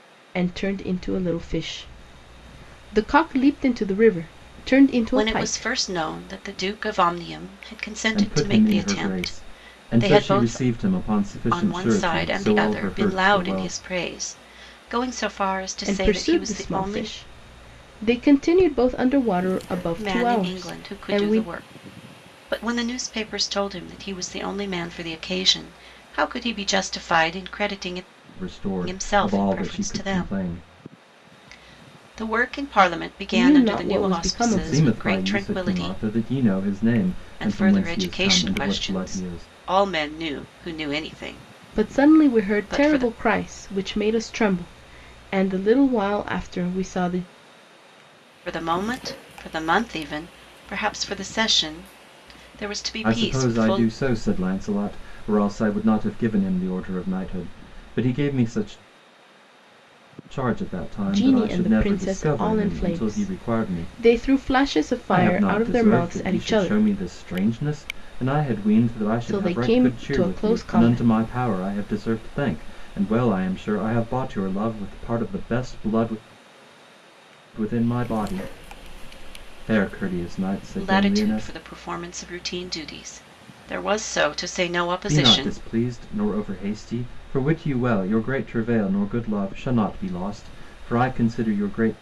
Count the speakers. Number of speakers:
3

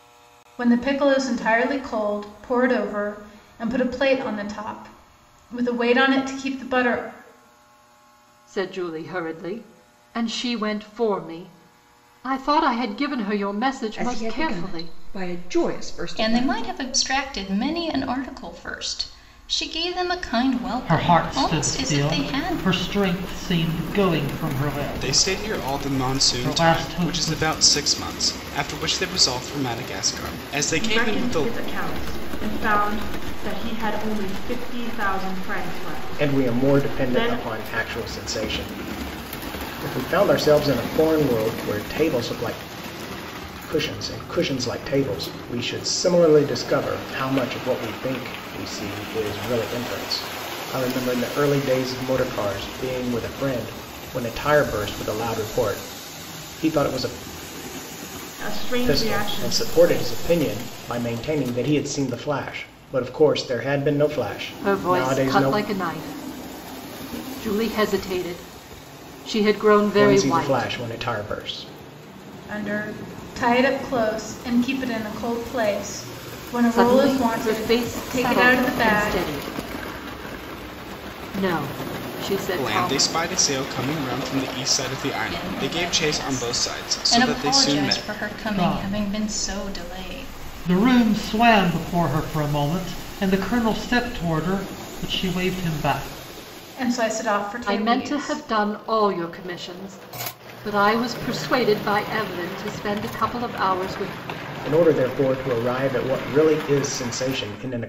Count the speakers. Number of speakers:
8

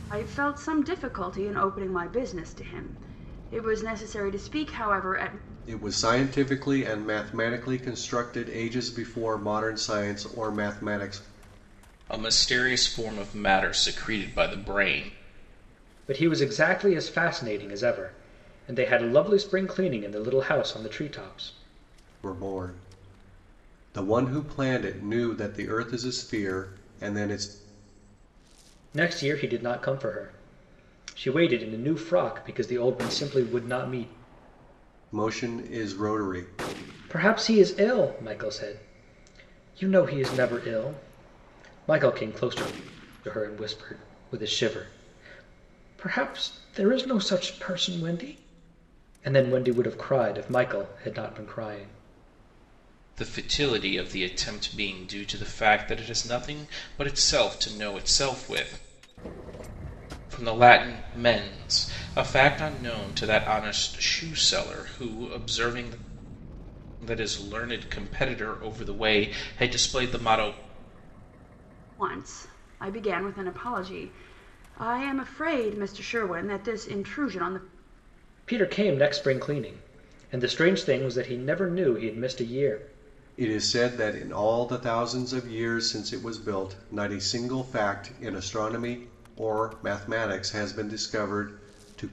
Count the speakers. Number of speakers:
4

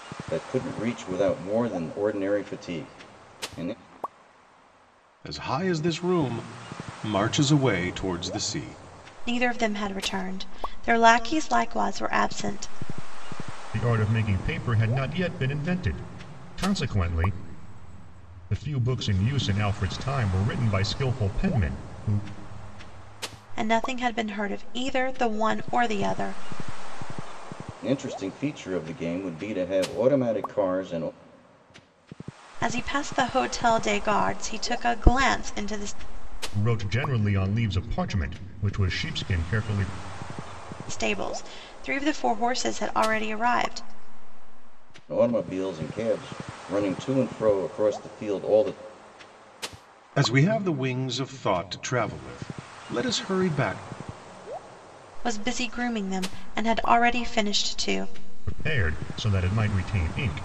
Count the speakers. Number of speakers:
4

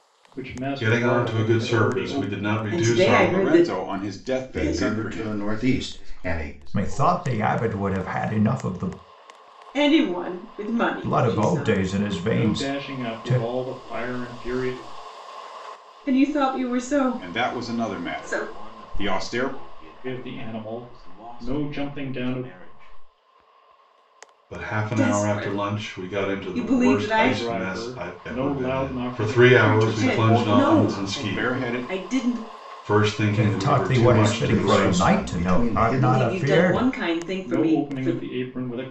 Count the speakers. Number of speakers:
7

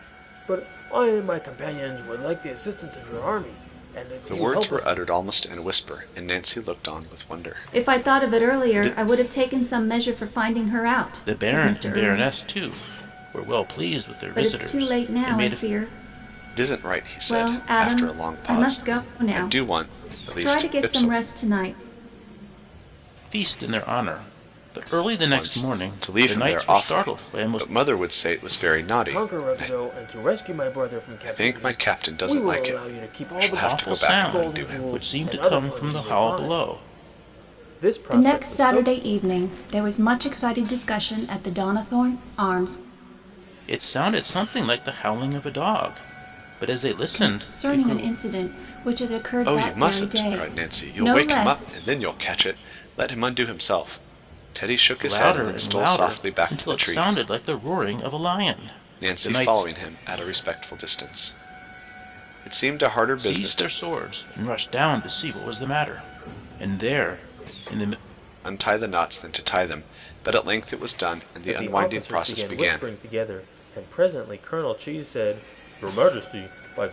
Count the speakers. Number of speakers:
4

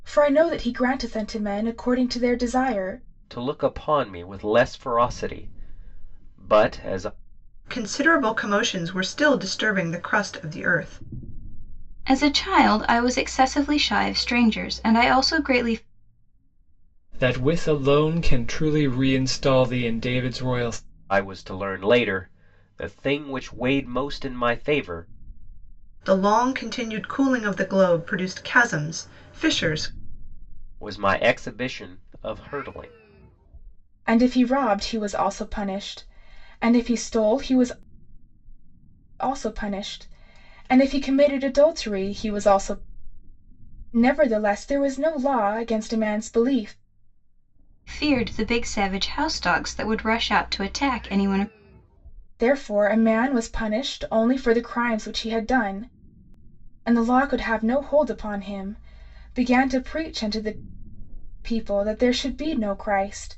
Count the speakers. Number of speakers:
5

